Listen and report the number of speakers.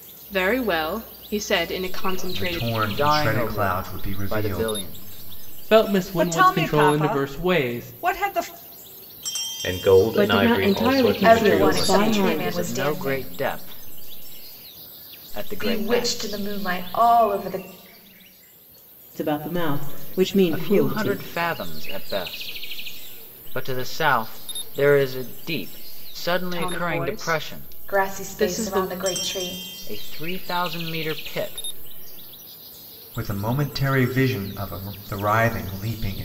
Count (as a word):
nine